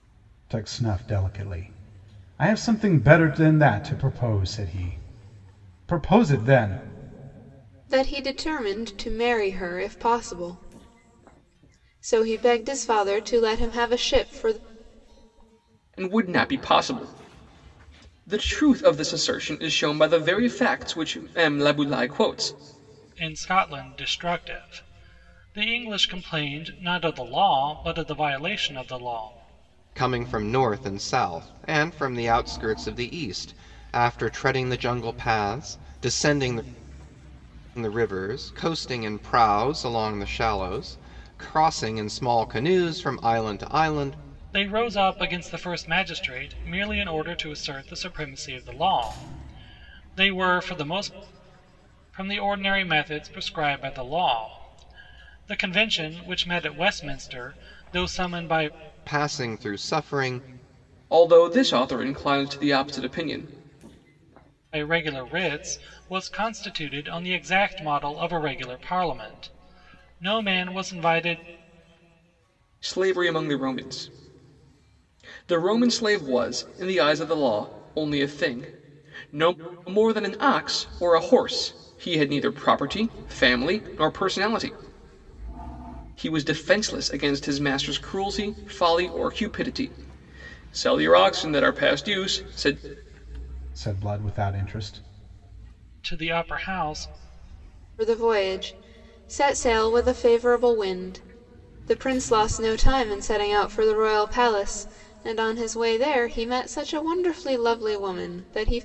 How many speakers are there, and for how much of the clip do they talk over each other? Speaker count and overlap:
5, no overlap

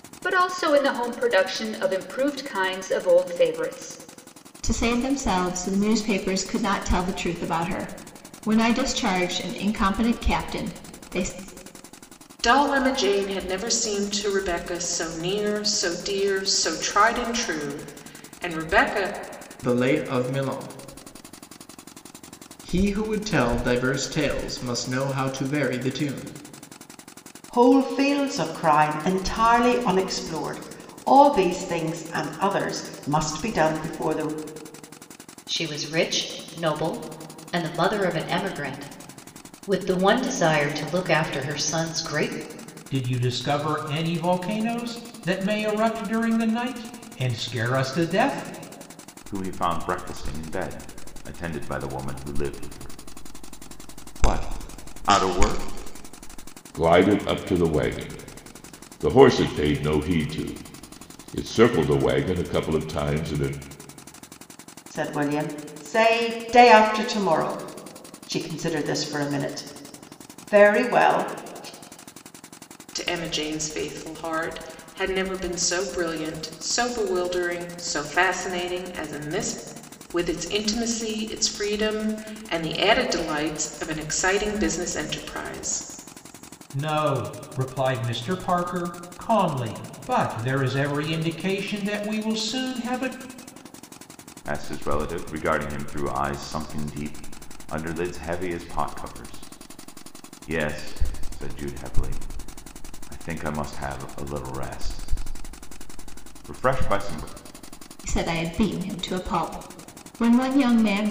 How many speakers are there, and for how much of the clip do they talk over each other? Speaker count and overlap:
9, no overlap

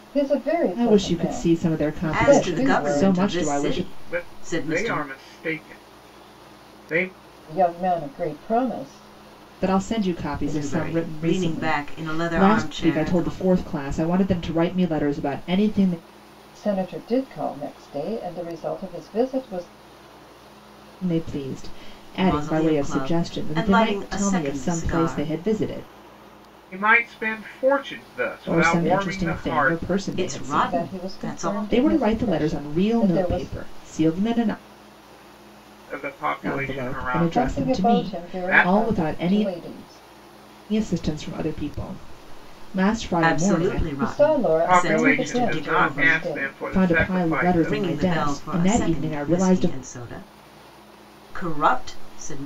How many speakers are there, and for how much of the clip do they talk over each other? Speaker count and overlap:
4, about 49%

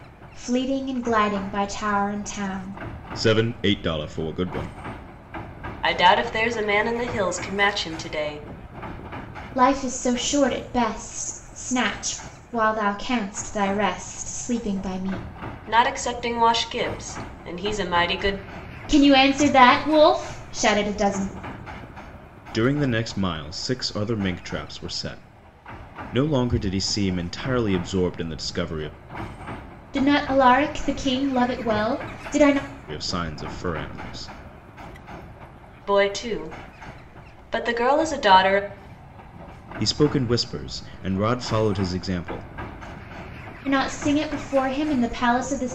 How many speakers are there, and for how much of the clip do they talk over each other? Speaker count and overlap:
3, no overlap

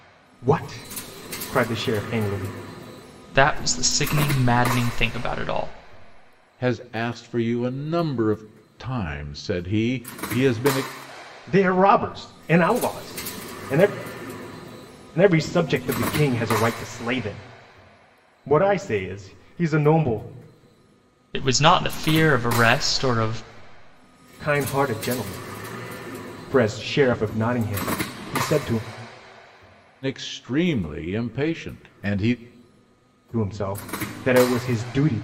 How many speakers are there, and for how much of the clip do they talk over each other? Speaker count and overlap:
3, no overlap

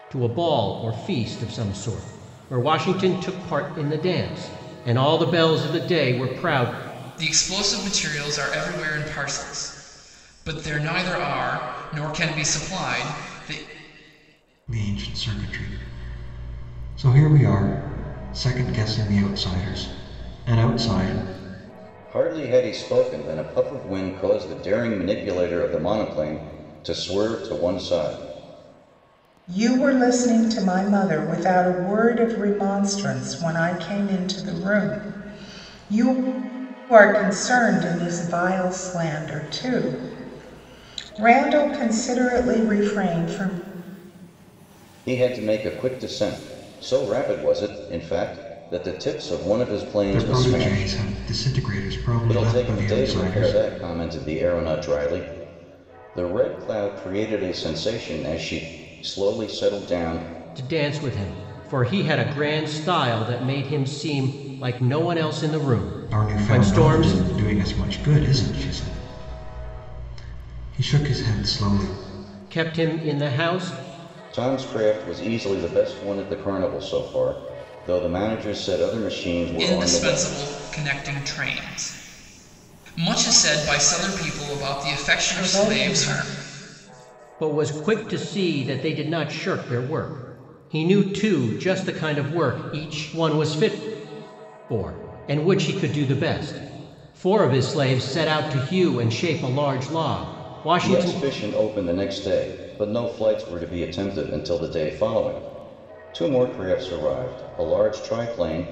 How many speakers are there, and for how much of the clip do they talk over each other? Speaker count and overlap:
5, about 5%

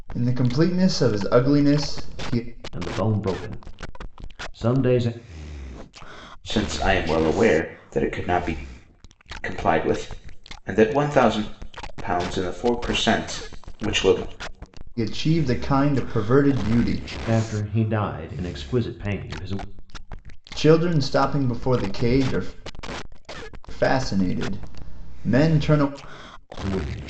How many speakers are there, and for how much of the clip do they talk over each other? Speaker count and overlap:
3, no overlap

